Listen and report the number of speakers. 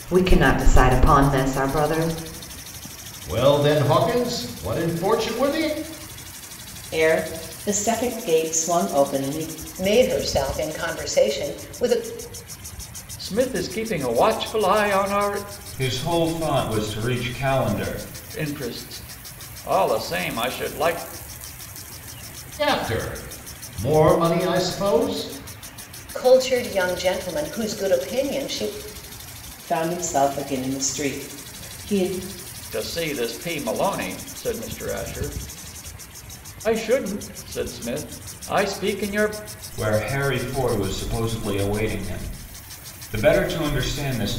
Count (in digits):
6